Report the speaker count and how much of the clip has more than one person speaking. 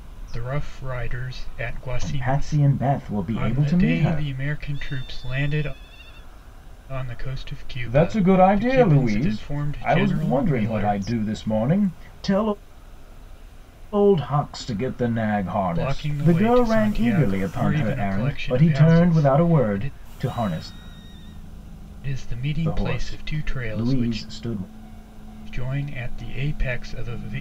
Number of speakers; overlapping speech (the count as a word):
two, about 39%